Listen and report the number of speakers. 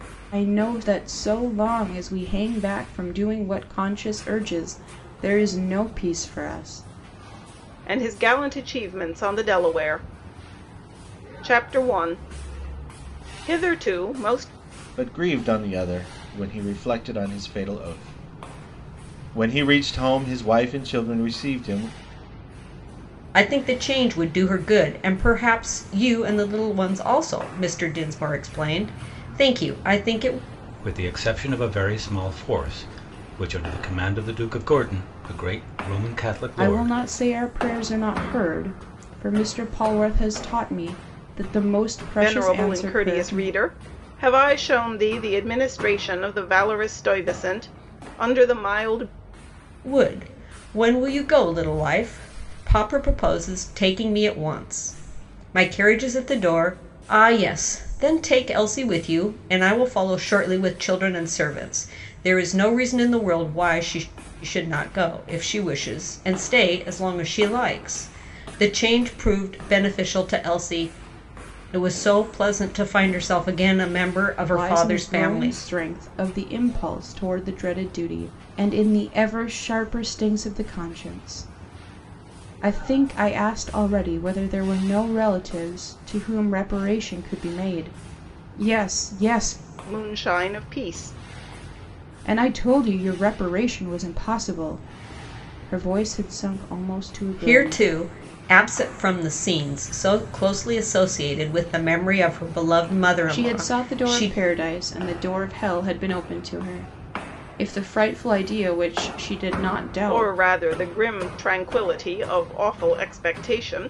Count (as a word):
five